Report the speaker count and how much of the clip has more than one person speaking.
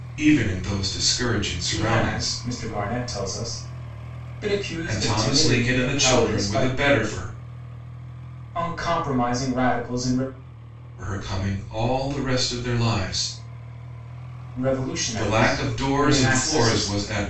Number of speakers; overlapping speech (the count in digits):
2, about 26%